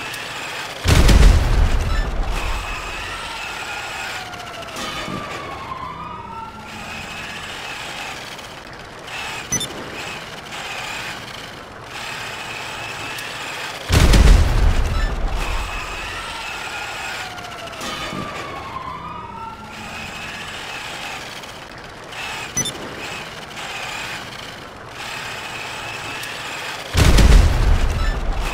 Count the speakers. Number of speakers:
0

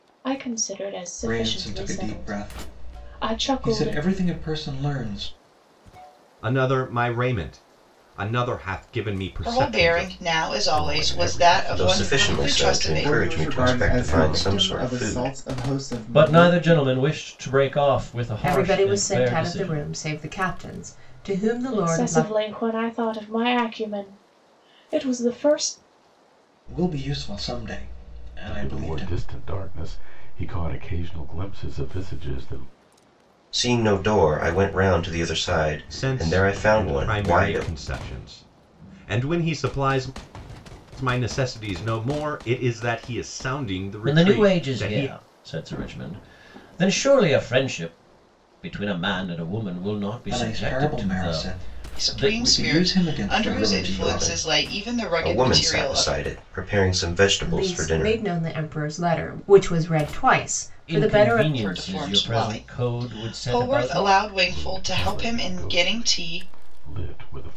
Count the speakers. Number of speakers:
9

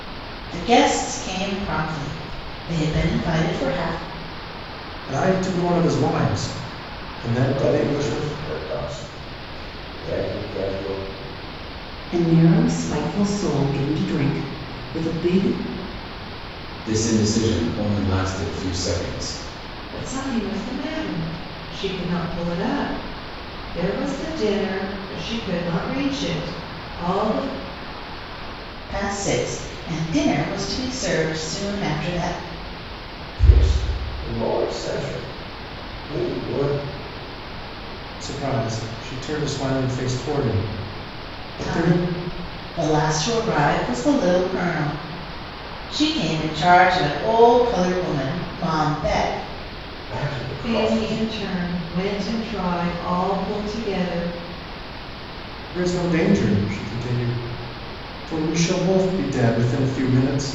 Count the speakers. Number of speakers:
6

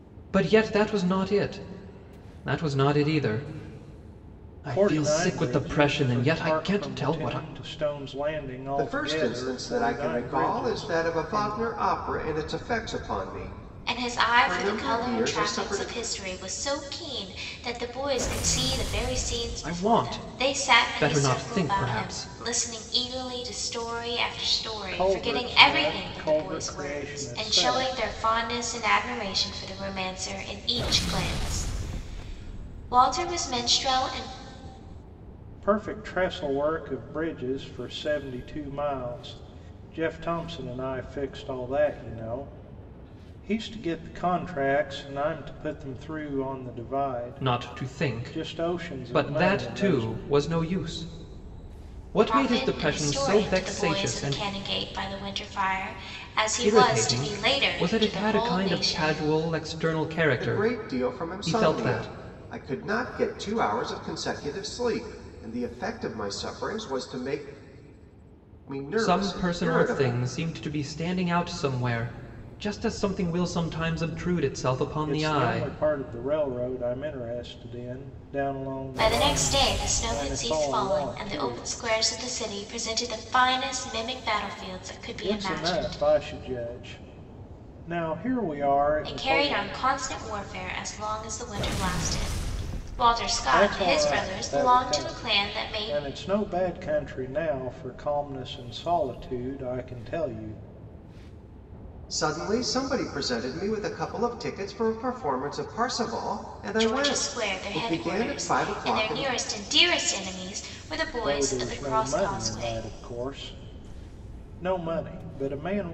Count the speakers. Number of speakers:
4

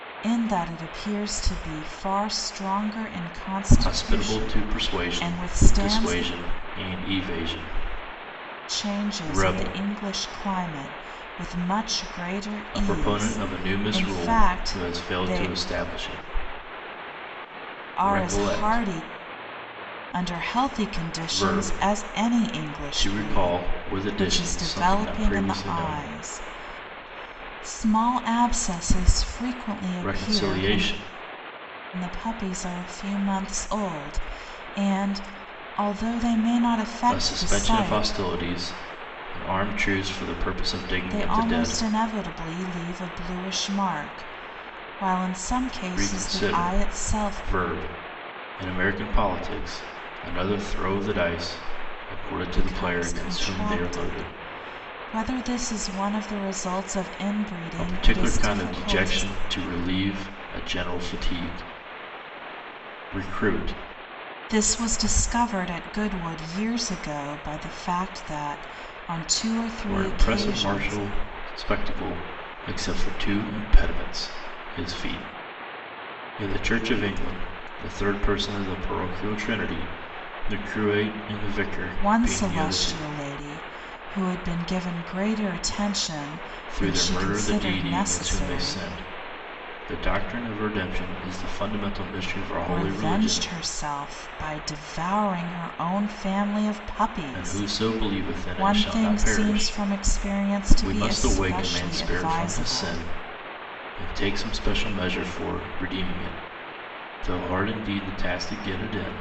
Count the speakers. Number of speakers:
2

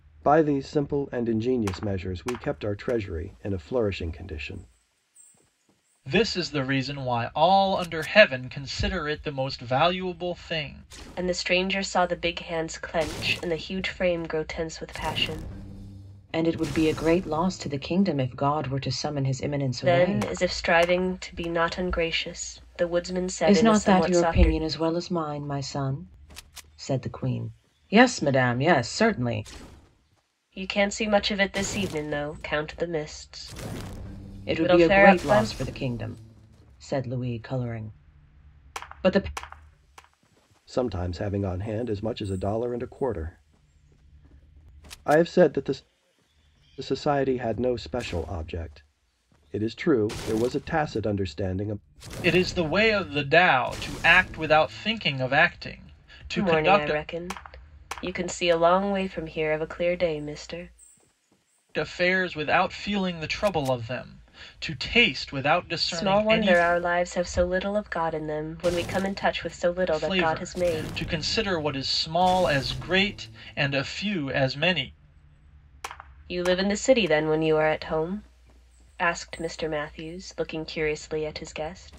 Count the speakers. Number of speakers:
4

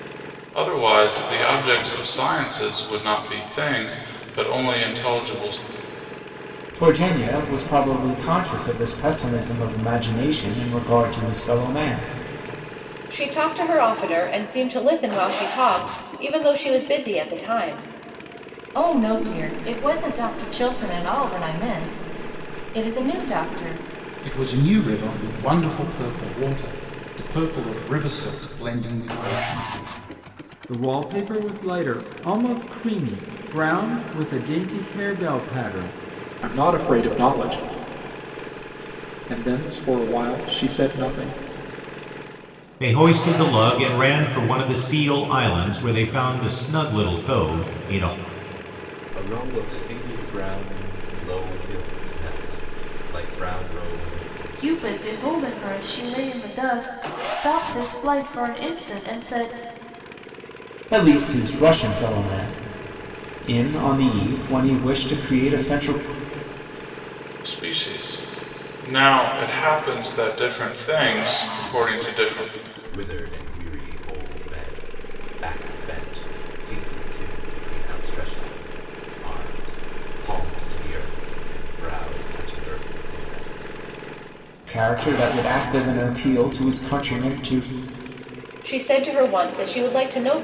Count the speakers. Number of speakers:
10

